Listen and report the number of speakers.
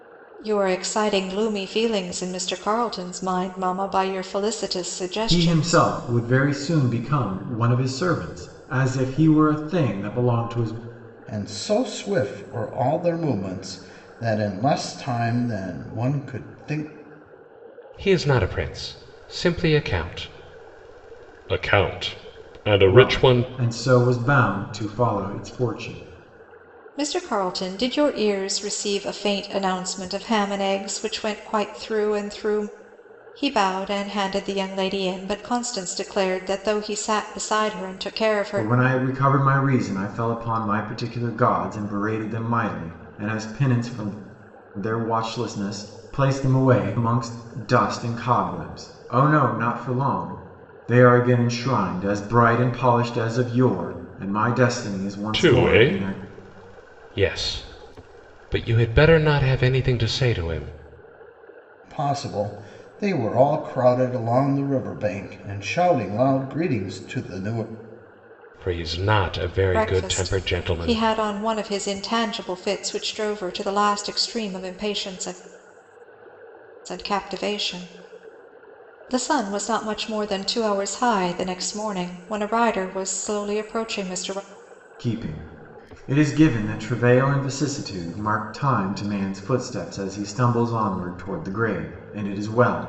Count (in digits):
4